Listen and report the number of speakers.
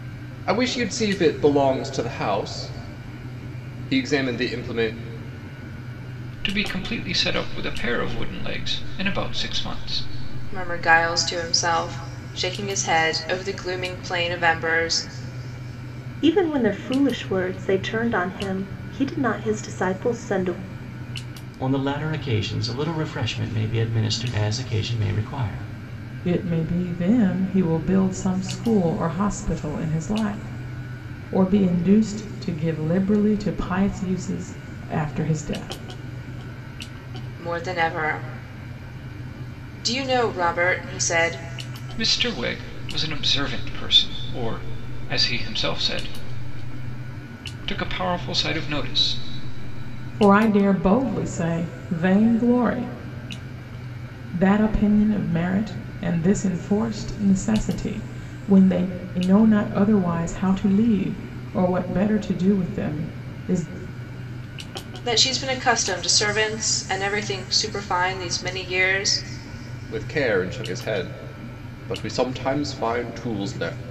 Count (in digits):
6